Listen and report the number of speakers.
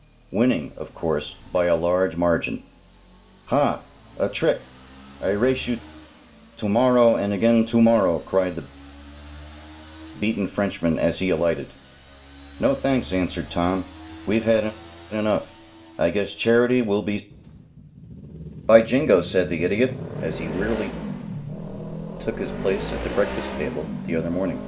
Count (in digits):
1